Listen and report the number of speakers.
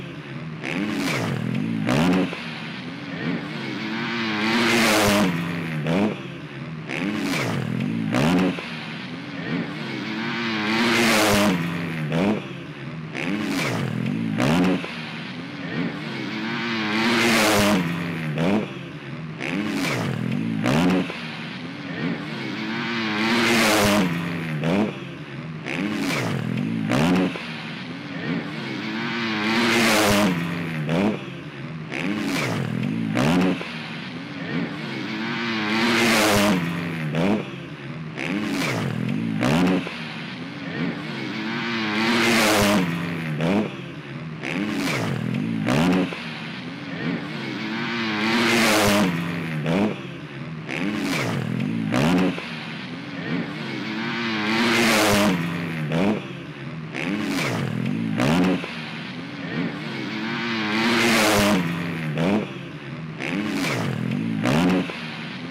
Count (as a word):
zero